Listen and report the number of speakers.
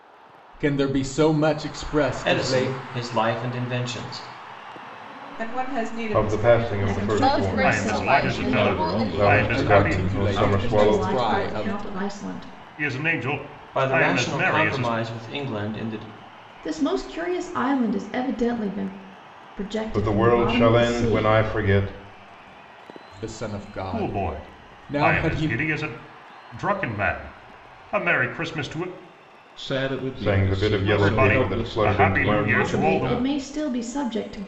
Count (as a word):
eight